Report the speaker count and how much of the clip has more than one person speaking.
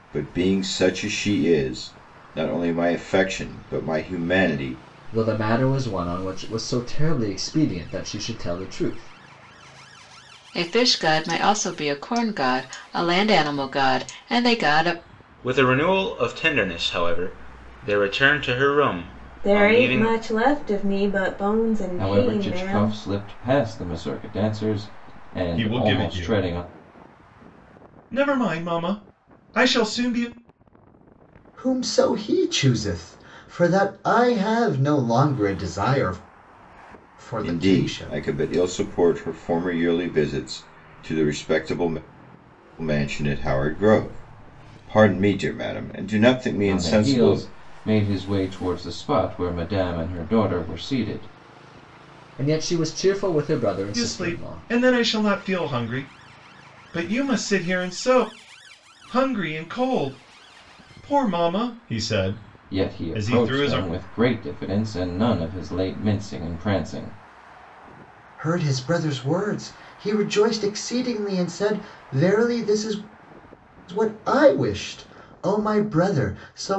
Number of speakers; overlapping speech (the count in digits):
8, about 8%